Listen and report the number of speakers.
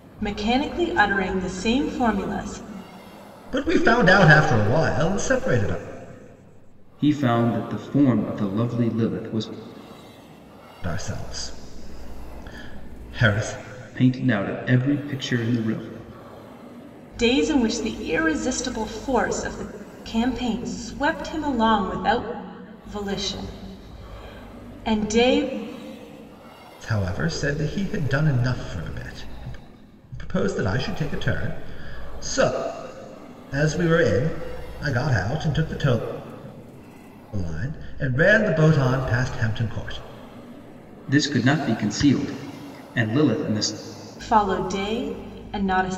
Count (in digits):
3